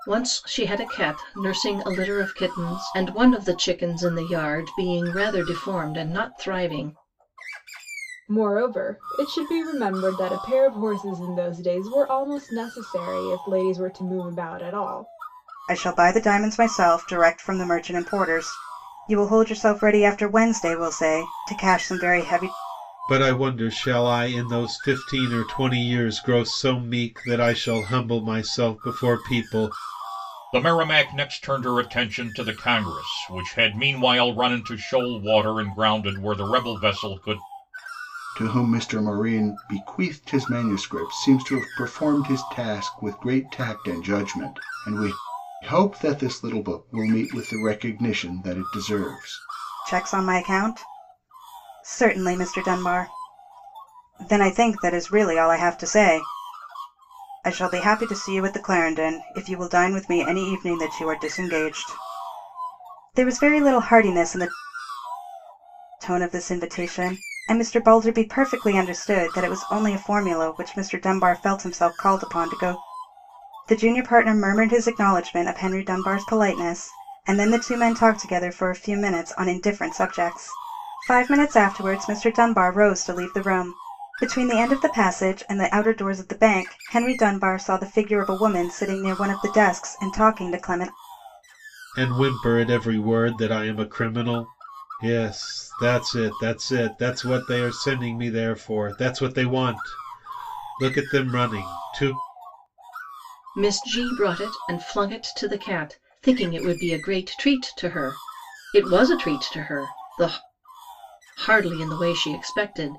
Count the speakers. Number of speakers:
six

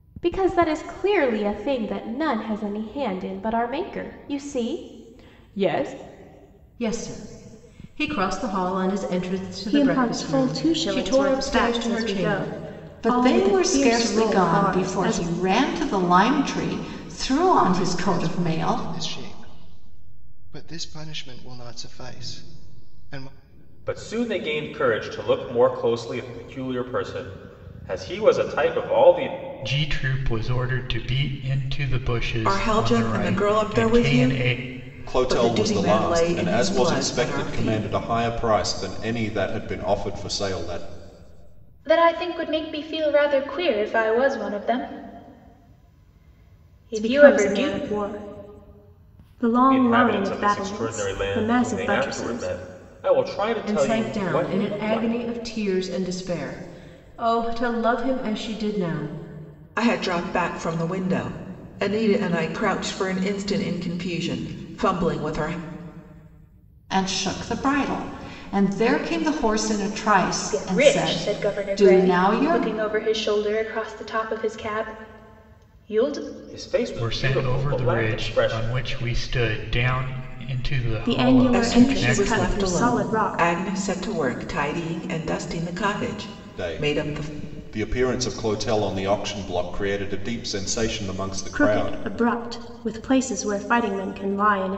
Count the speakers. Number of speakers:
ten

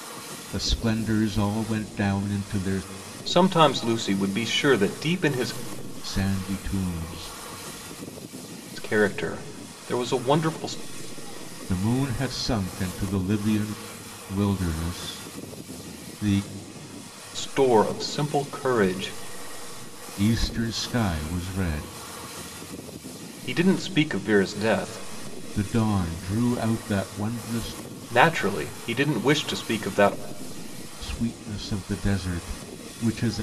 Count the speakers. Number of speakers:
two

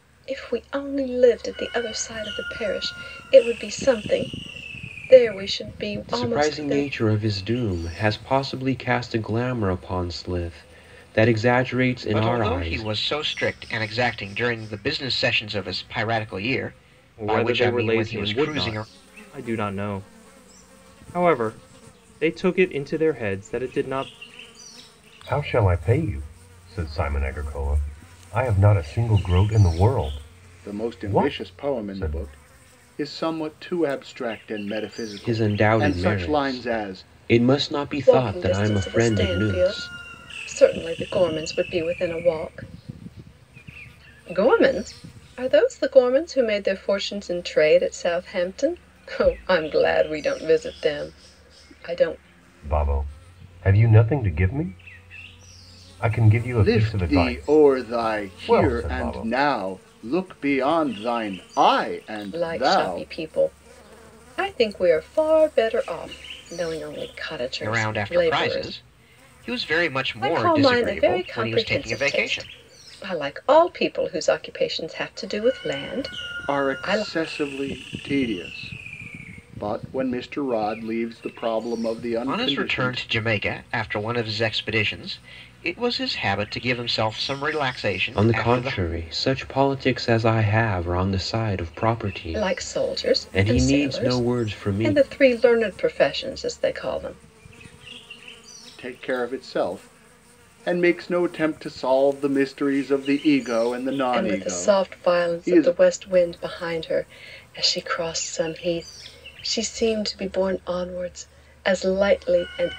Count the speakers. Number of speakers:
six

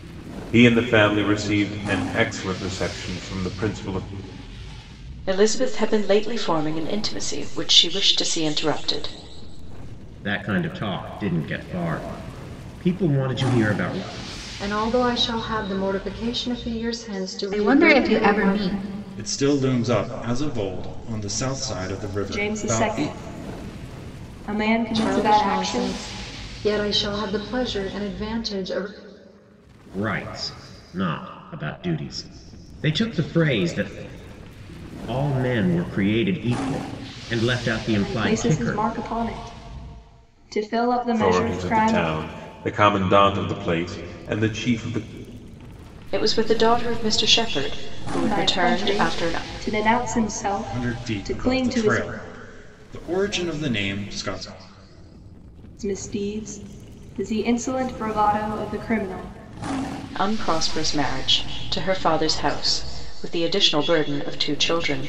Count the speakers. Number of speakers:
seven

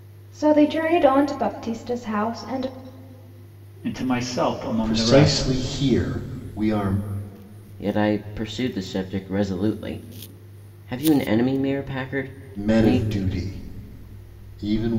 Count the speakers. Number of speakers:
four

